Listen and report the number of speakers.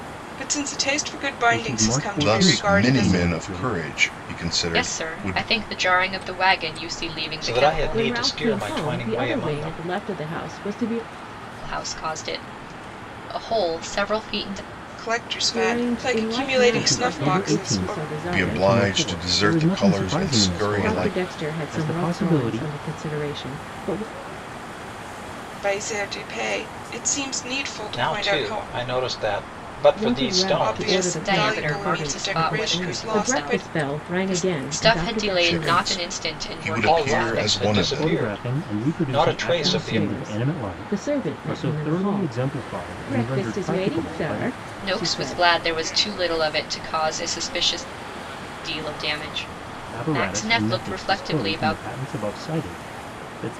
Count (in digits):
6